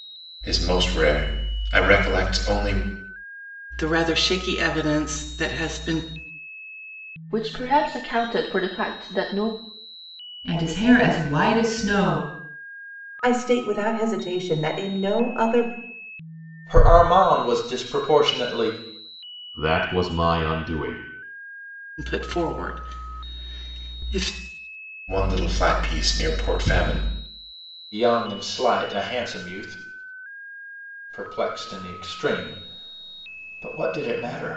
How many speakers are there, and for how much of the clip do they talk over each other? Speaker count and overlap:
7, no overlap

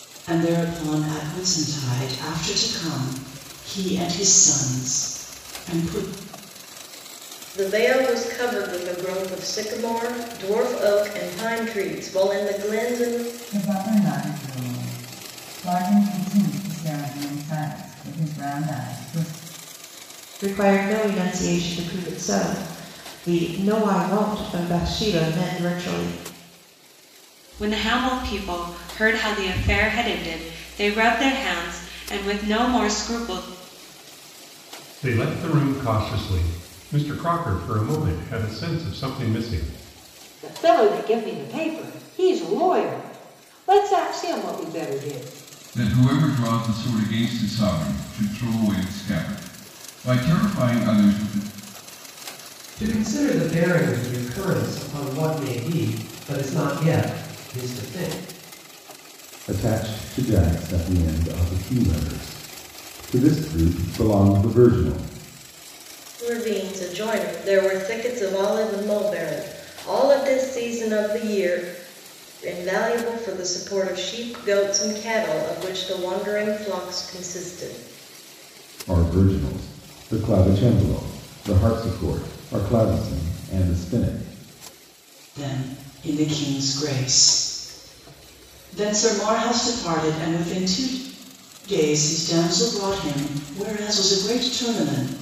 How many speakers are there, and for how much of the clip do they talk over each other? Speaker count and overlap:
10, no overlap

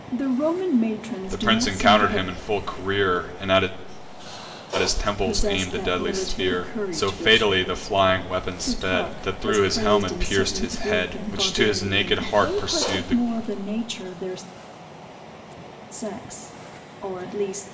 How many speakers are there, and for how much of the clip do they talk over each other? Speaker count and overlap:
2, about 45%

